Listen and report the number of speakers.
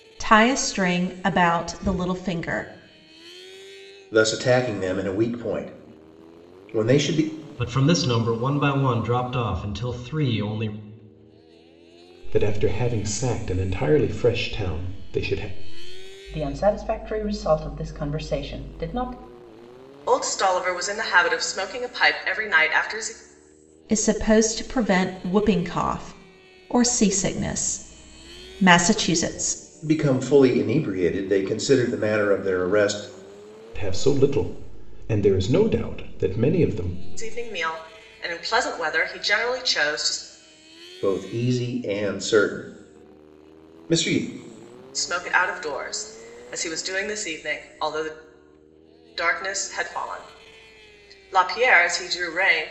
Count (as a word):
six